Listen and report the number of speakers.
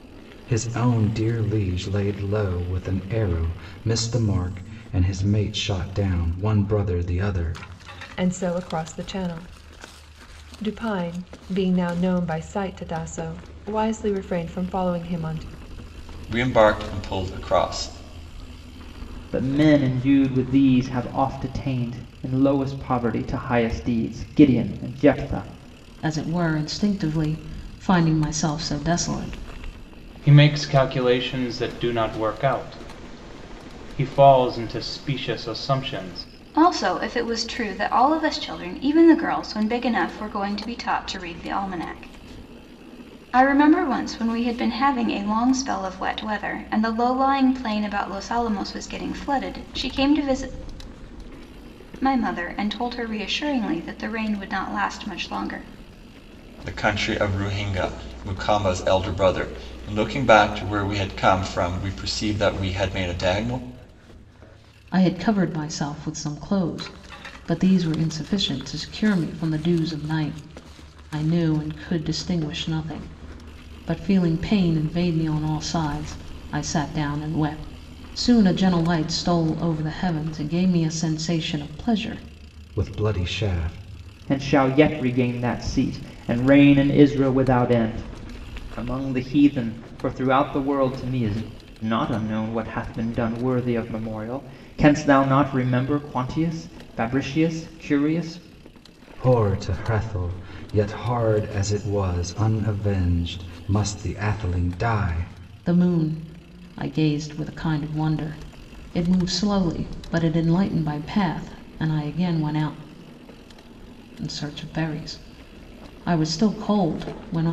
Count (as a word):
seven